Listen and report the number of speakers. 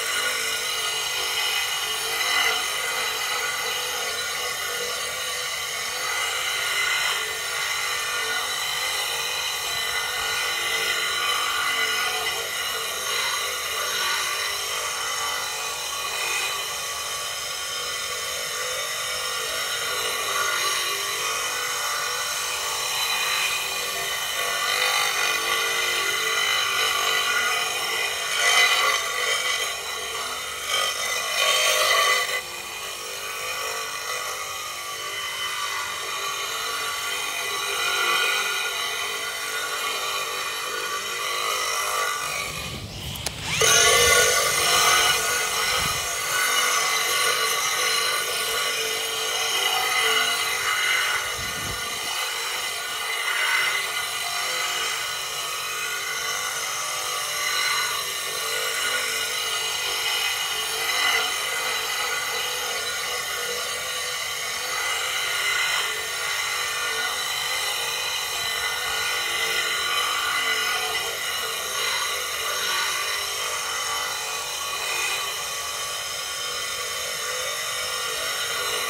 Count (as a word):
zero